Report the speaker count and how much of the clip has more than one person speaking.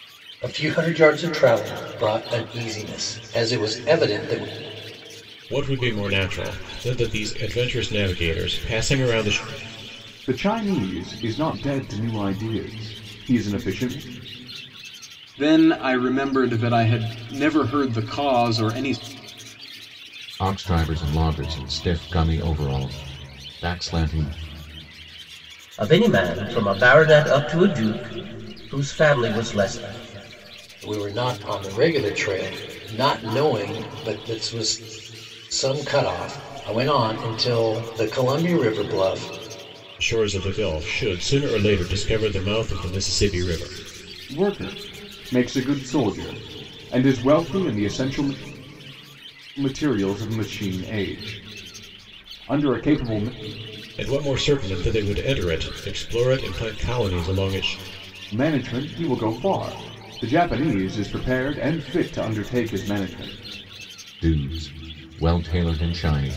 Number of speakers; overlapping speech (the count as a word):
six, no overlap